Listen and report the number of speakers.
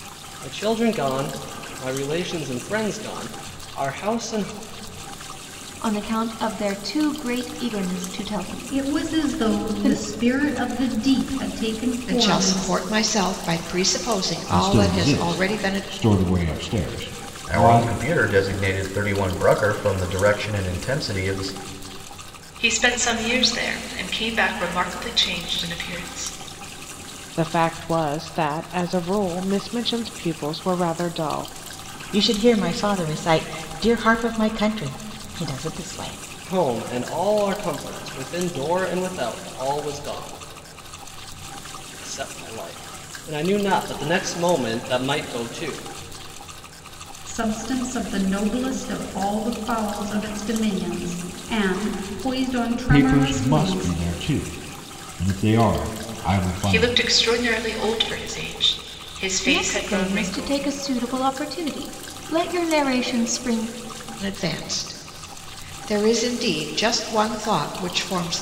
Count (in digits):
9